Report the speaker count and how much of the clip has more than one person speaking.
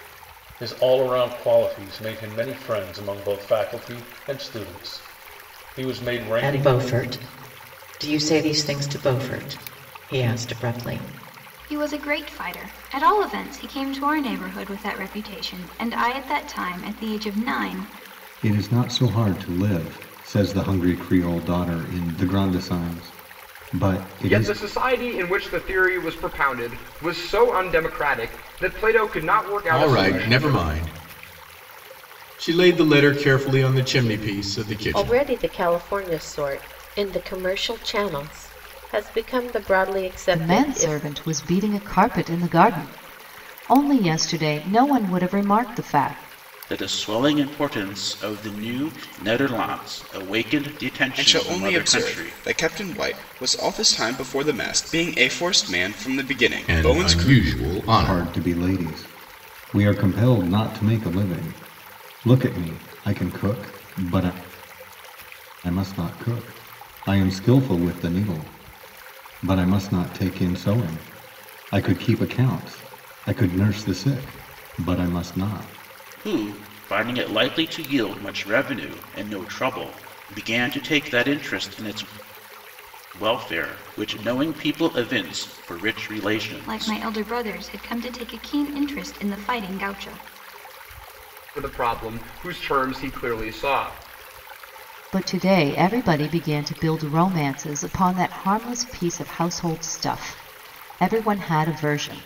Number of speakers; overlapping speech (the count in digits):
10, about 5%